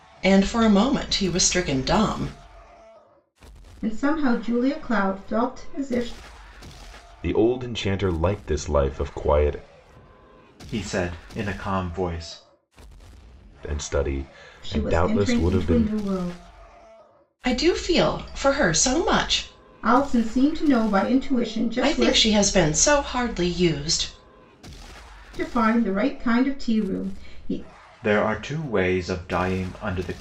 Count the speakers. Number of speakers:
4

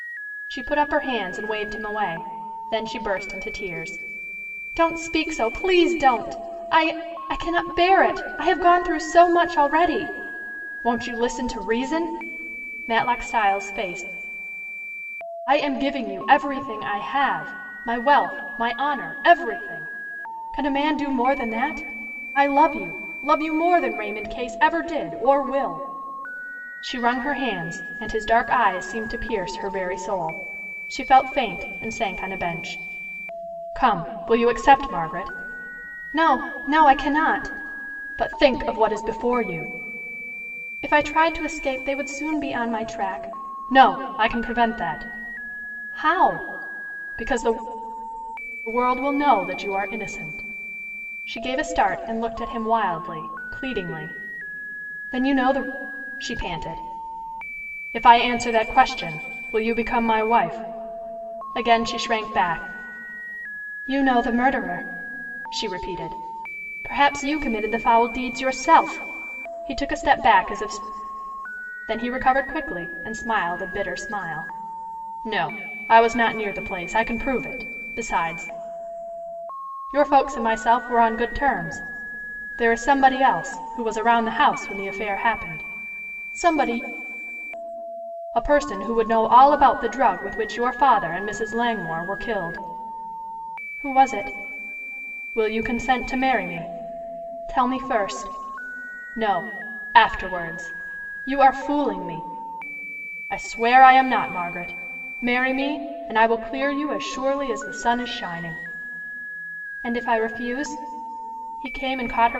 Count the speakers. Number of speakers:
1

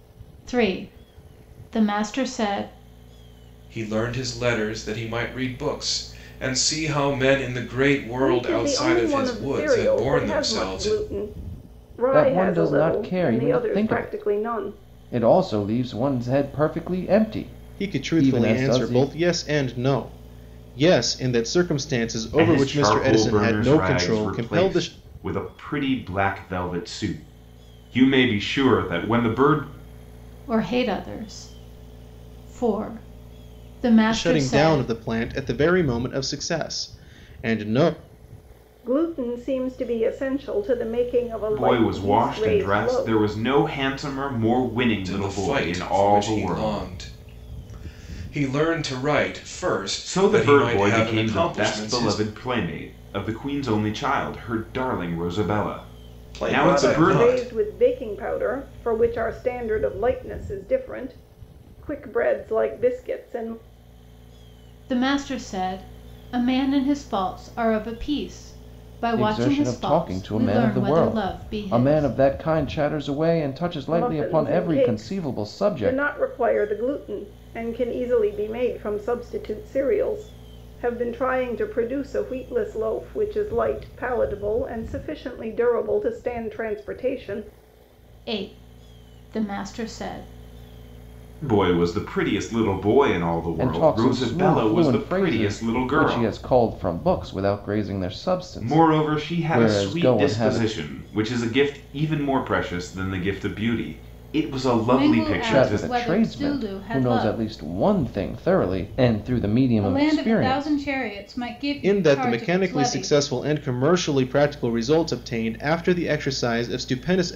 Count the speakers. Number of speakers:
6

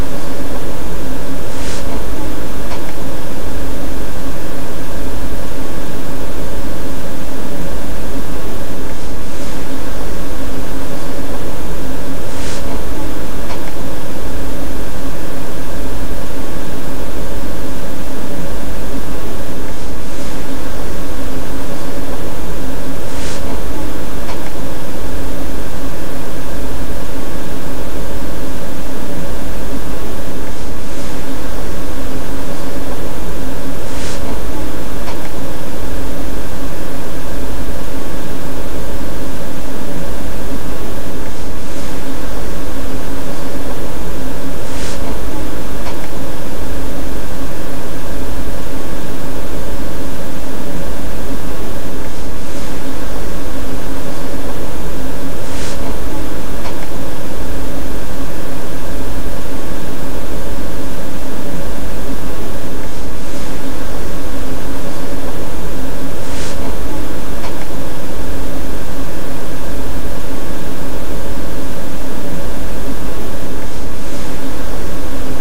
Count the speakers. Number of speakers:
0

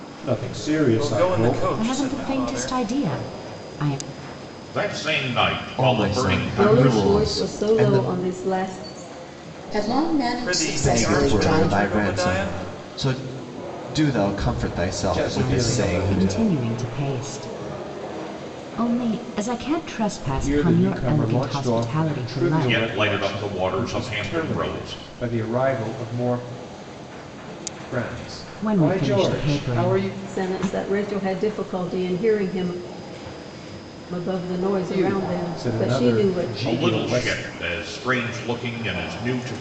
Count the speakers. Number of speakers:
7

